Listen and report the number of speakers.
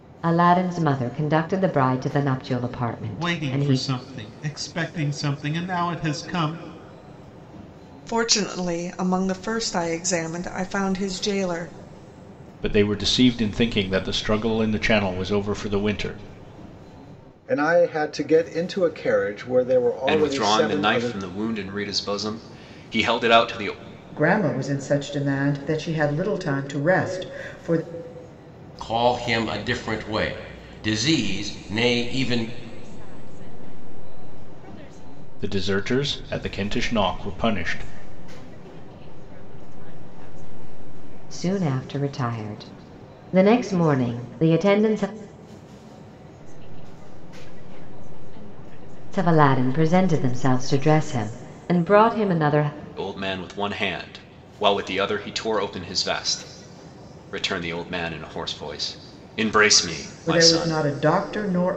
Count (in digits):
9